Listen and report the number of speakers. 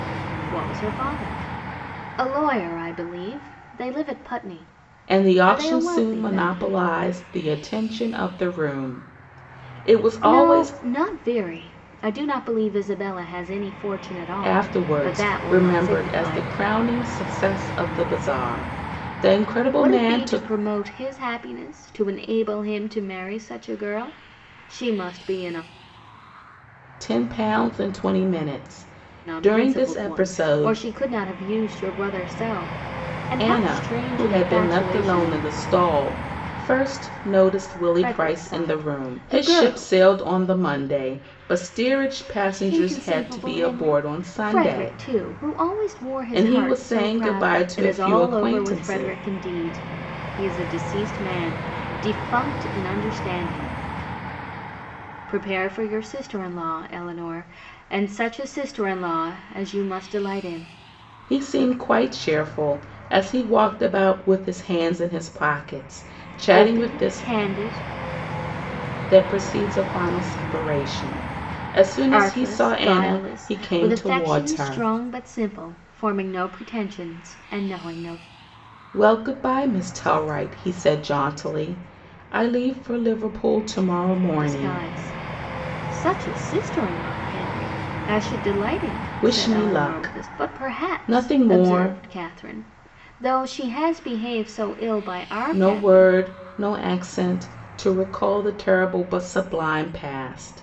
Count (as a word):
two